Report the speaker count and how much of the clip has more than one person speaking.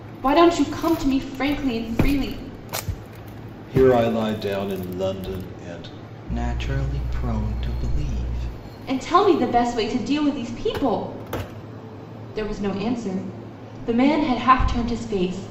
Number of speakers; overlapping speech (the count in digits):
3, no overlap